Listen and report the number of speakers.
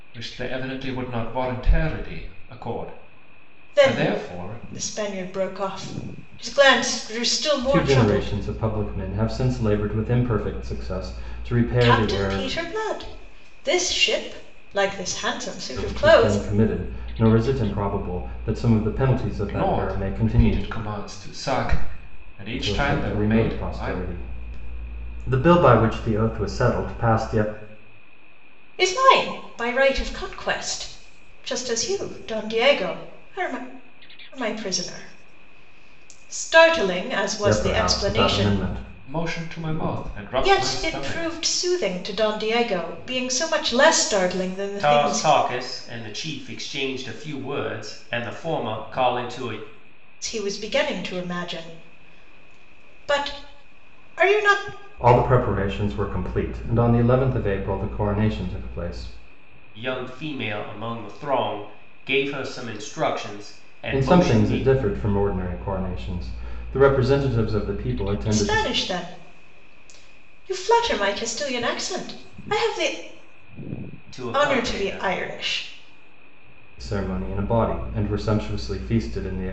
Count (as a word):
three